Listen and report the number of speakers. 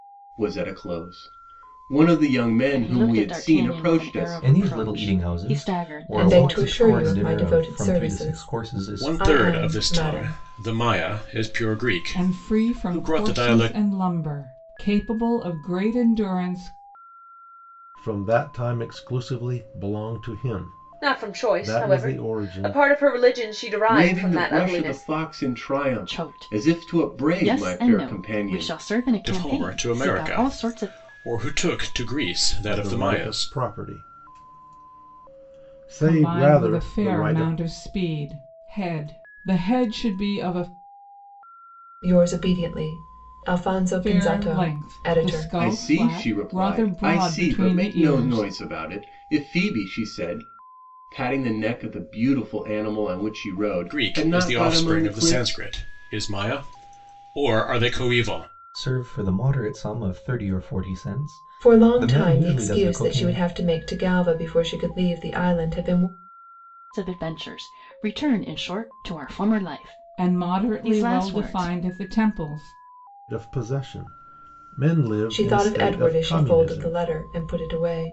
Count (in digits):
8